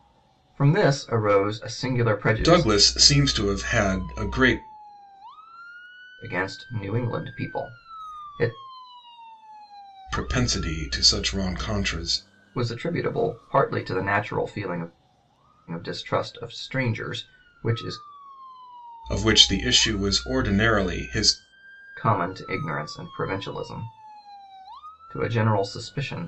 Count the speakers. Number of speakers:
2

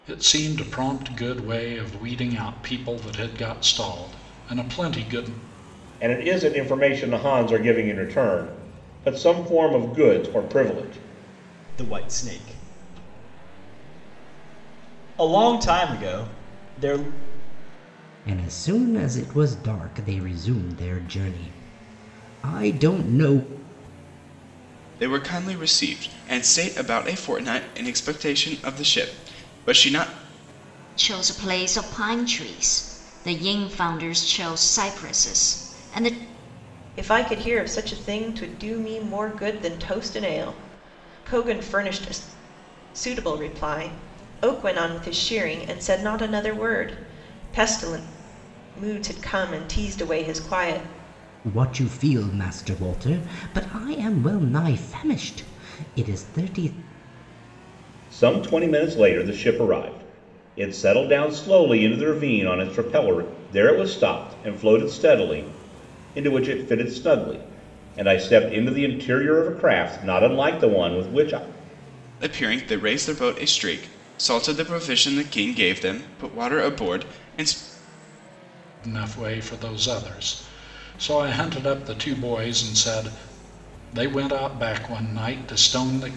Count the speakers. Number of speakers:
7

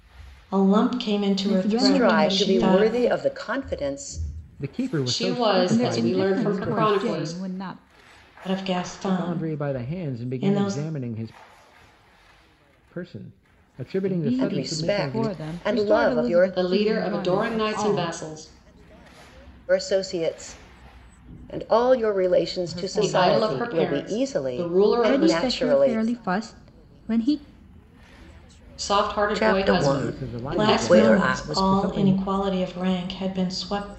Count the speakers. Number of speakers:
6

